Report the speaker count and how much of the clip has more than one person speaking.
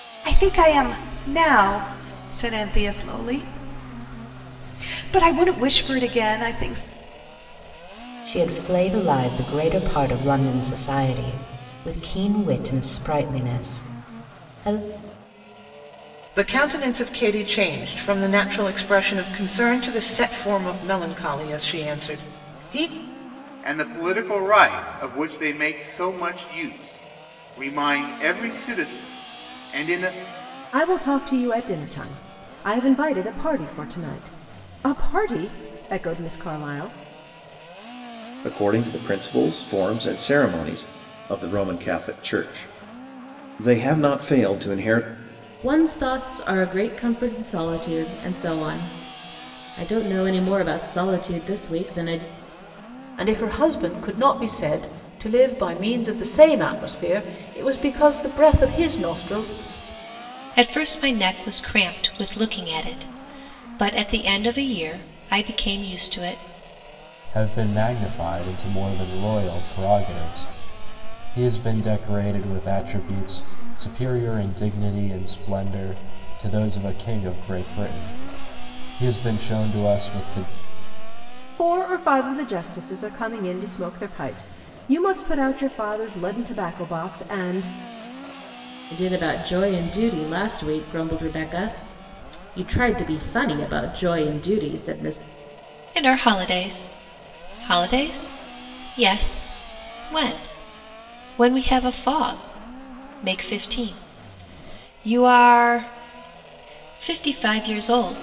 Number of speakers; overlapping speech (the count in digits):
10, no overlap